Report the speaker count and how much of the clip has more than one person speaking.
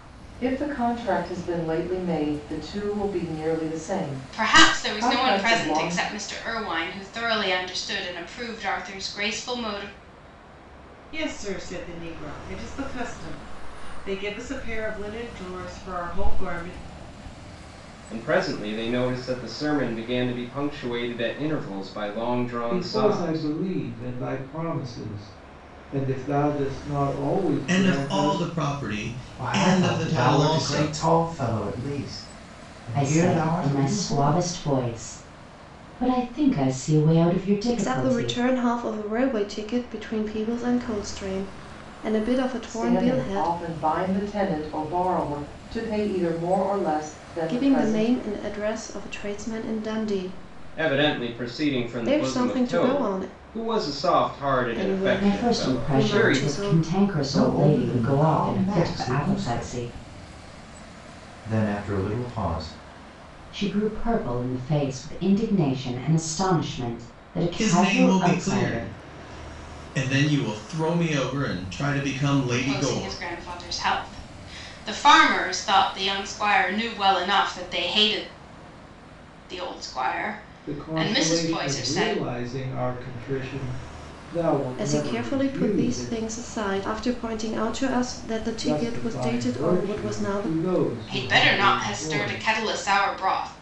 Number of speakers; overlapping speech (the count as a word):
nine, about 27%